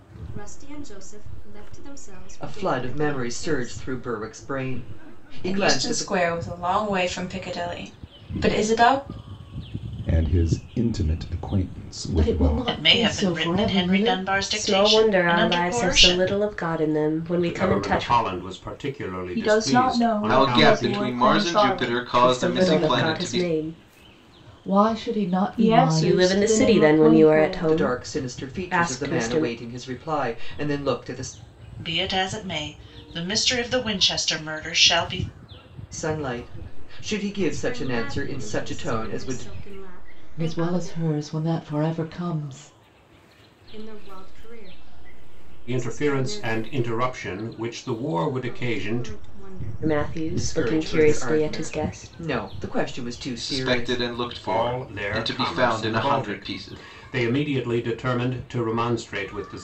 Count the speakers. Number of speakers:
ten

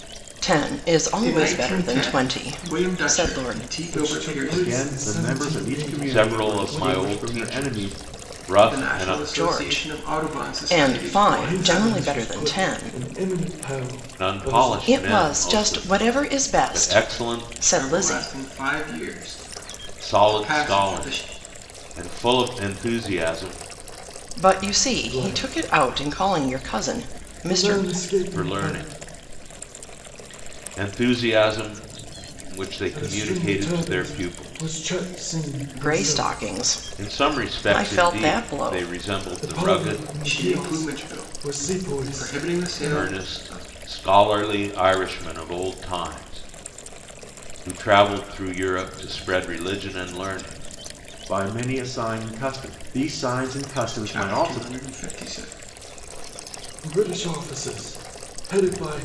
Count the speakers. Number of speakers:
five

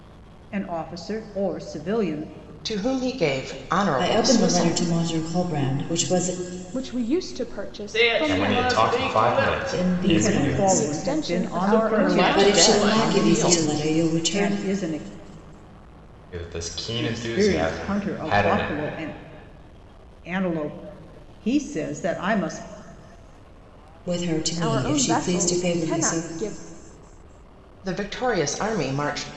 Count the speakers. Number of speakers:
six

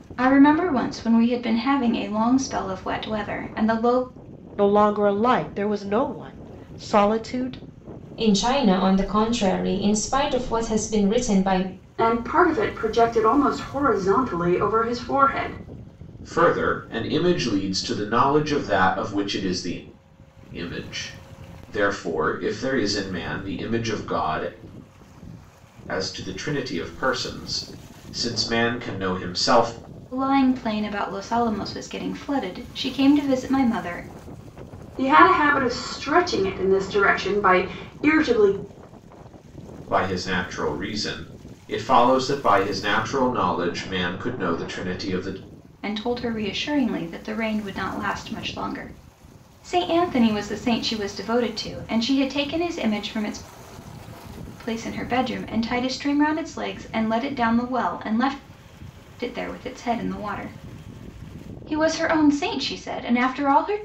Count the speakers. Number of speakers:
five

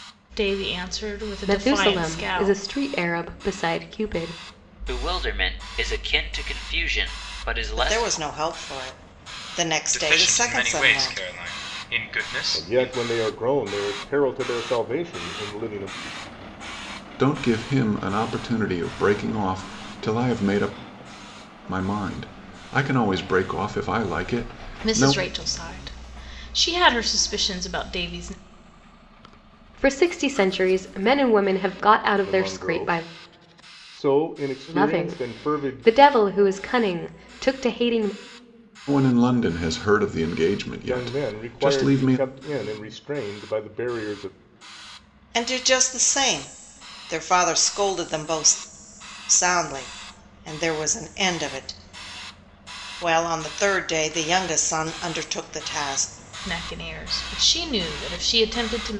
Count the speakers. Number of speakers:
seven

